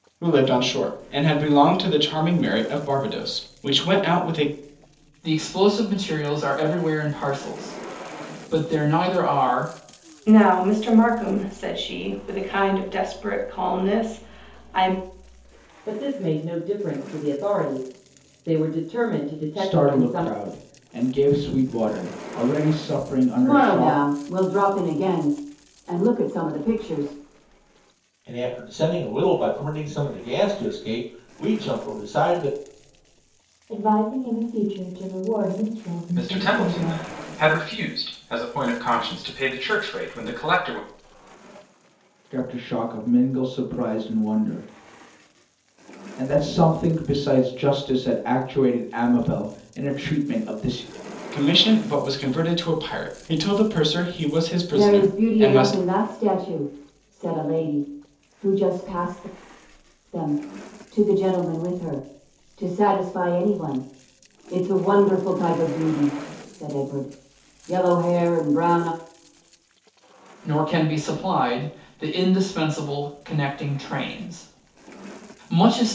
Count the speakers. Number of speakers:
nine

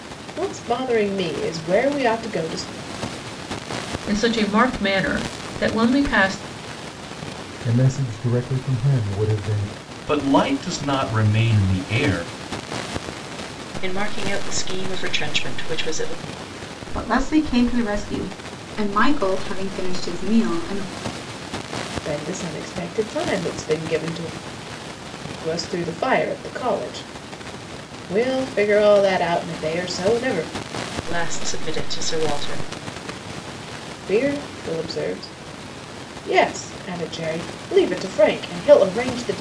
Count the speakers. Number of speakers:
seven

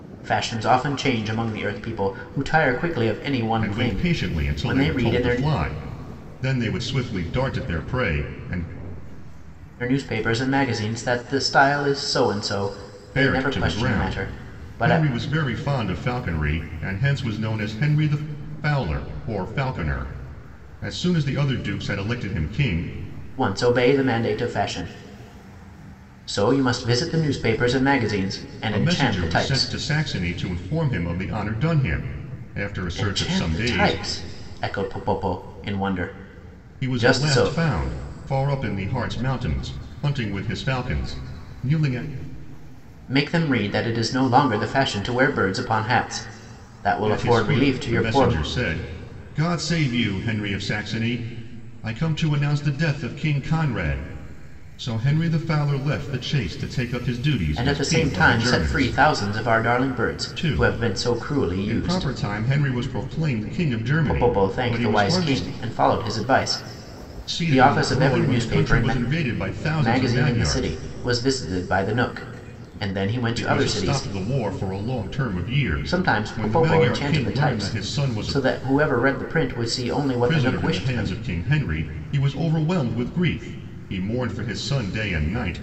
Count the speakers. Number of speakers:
two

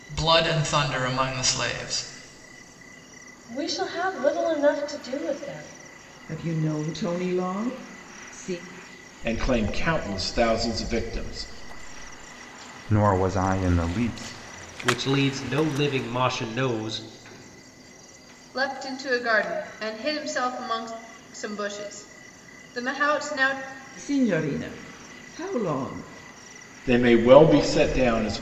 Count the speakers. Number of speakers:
seven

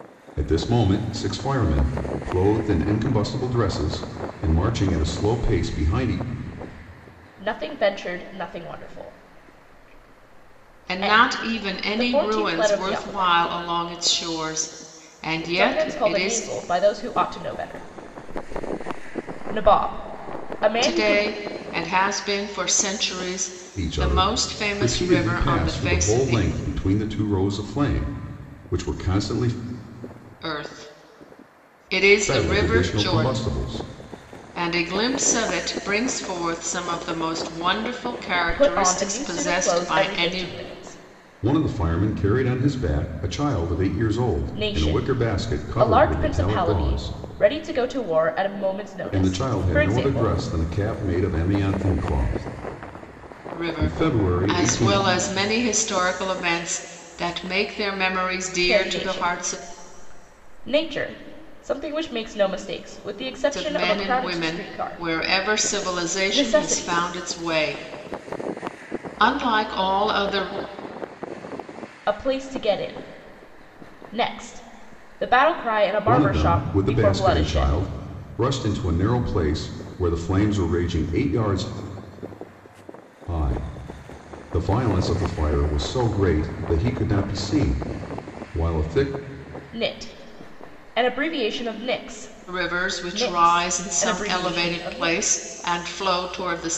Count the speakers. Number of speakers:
three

